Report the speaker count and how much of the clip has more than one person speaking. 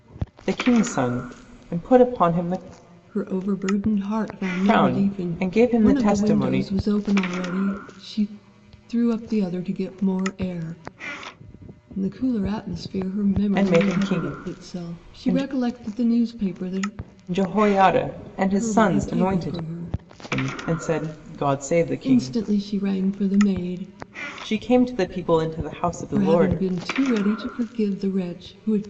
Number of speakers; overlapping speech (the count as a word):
two, about 19%